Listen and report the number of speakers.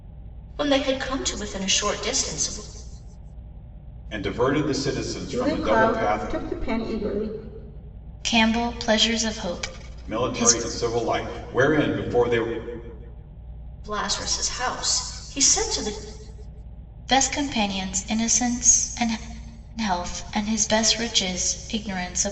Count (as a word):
four